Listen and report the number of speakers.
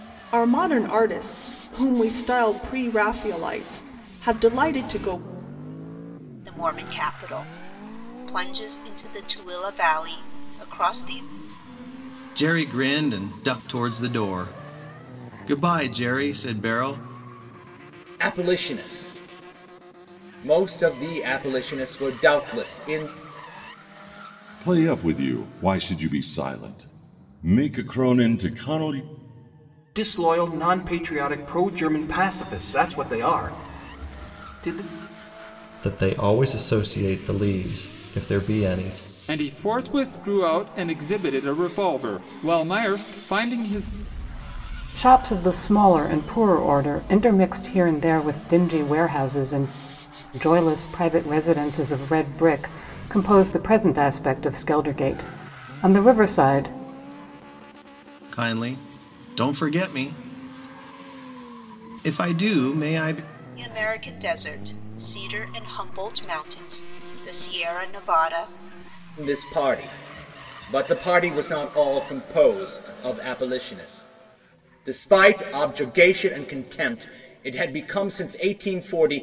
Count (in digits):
9